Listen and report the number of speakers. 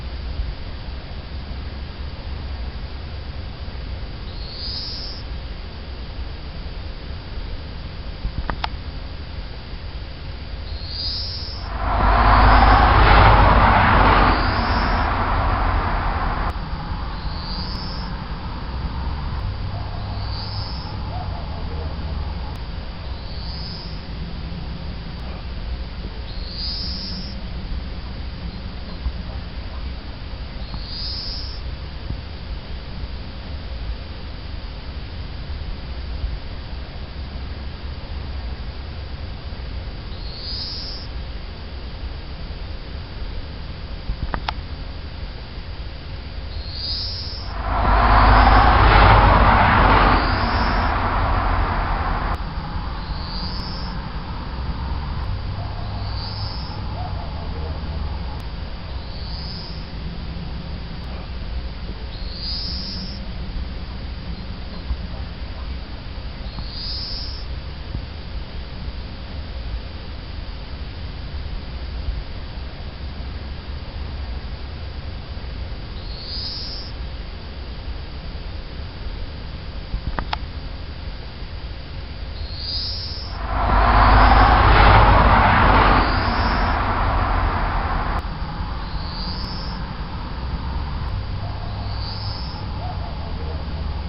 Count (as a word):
zero